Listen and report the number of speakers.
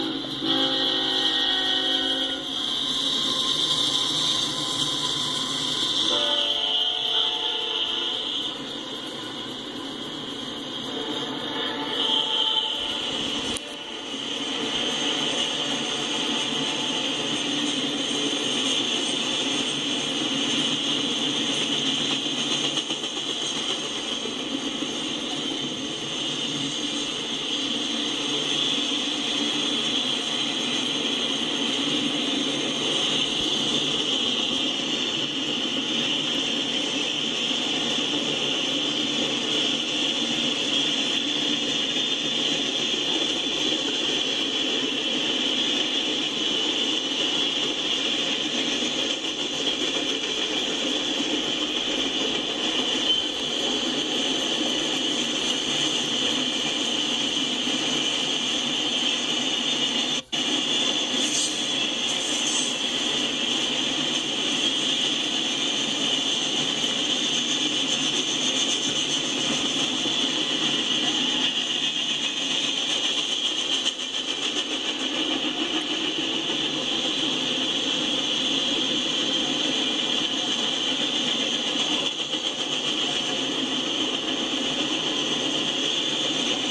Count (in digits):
0